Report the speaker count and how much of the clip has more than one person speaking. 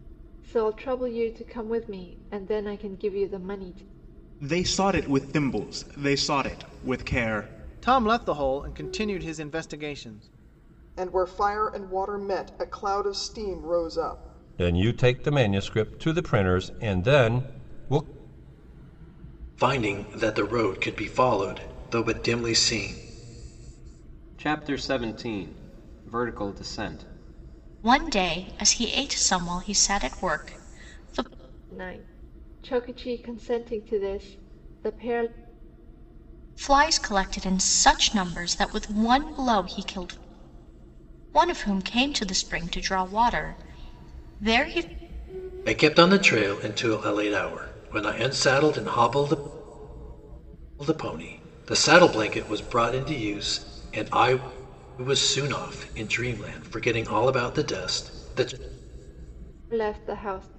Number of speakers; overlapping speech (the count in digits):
8, no overlap